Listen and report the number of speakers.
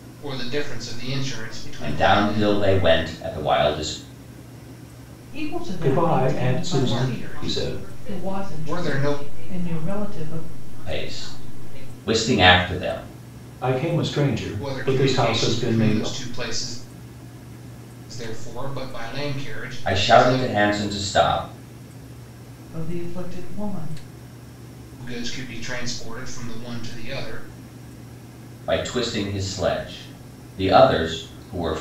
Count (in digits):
5